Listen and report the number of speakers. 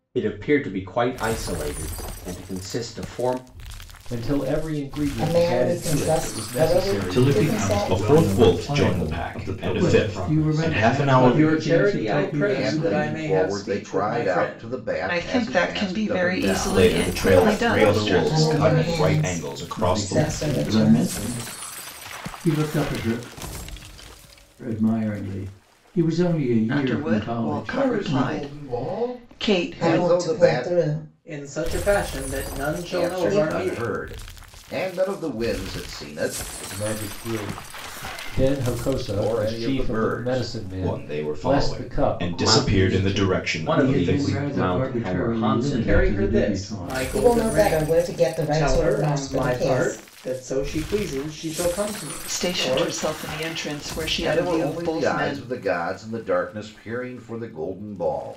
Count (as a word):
nine